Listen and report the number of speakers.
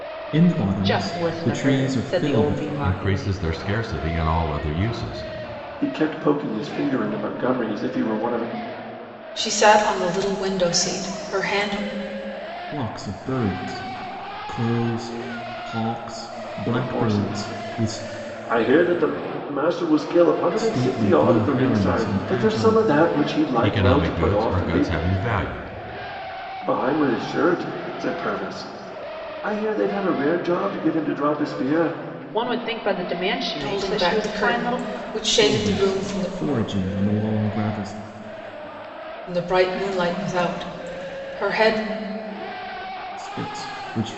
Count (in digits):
5